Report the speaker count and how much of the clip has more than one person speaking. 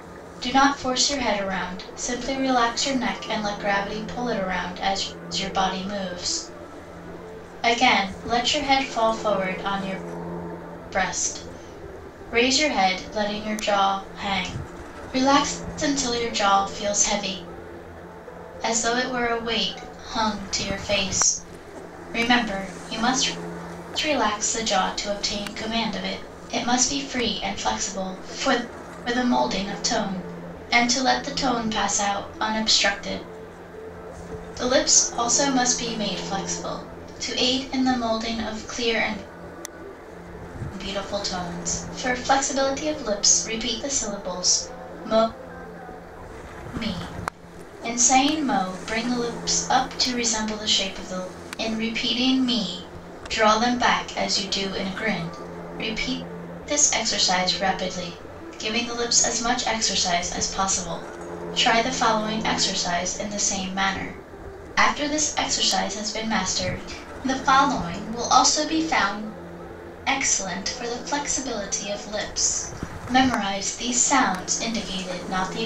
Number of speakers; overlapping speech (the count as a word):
one, no overlap